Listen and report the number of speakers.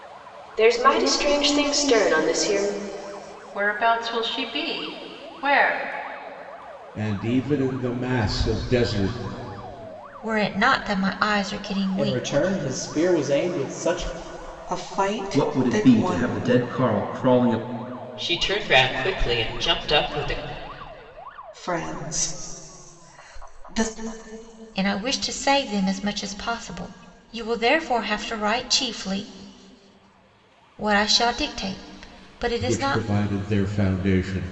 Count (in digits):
8